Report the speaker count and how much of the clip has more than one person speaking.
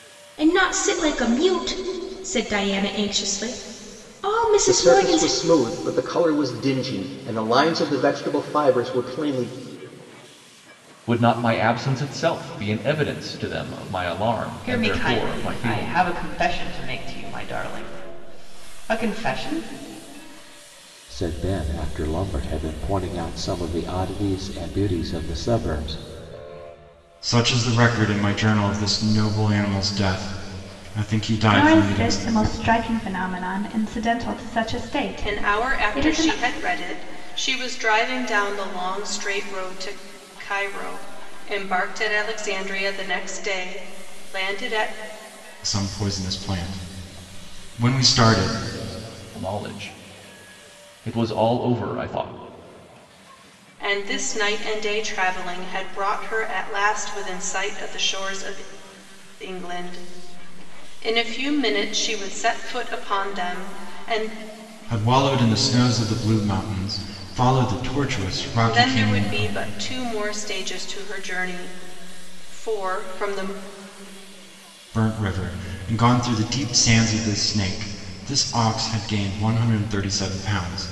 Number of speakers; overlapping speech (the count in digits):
8, about 6%